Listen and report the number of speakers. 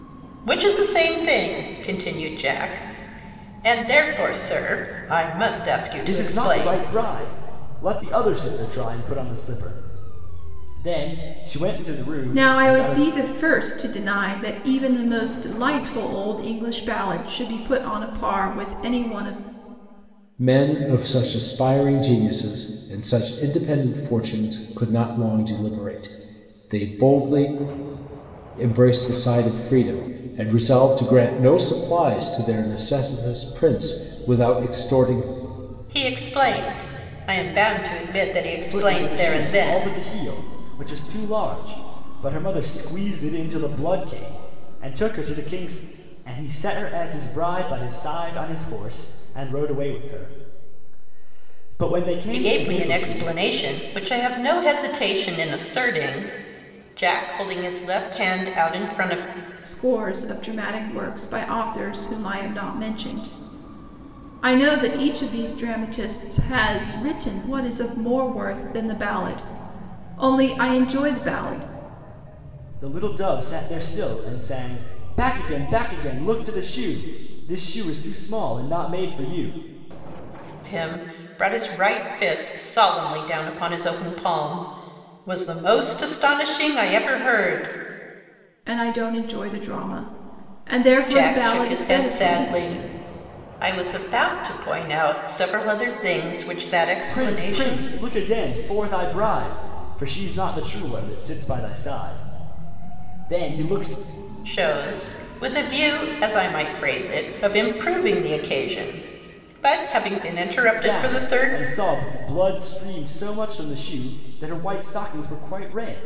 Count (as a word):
four